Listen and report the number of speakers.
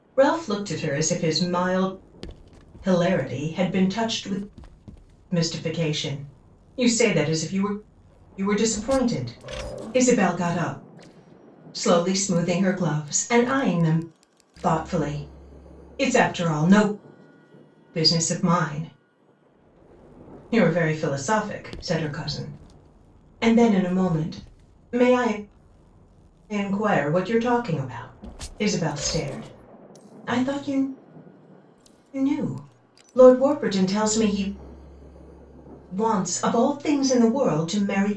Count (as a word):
one